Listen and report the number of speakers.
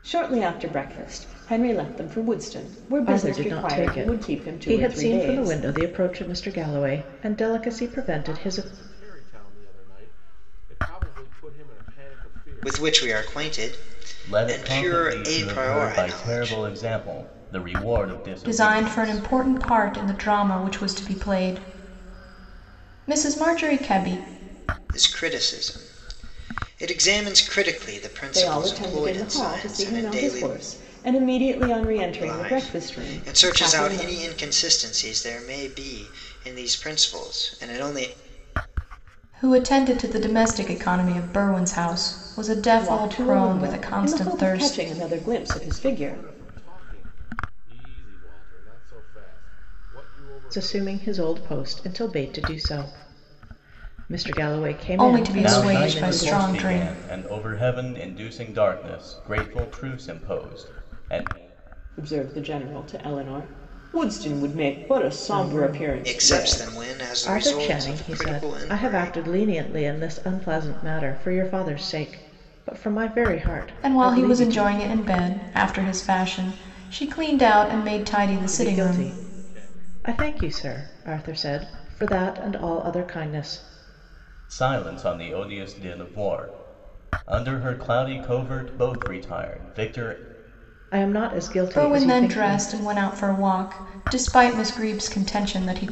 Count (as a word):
six